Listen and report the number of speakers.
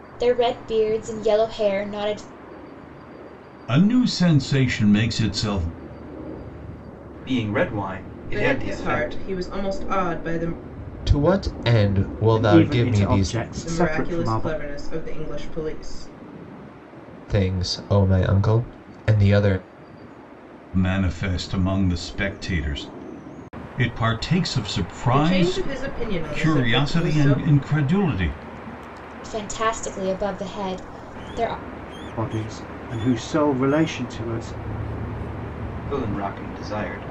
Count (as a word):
six